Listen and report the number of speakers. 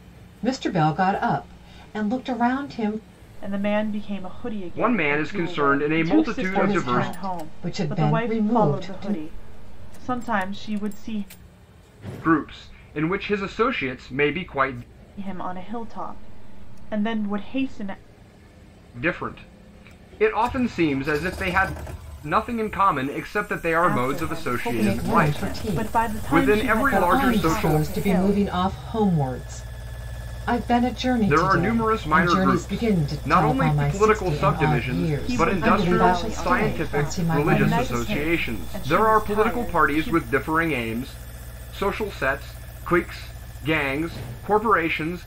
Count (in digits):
3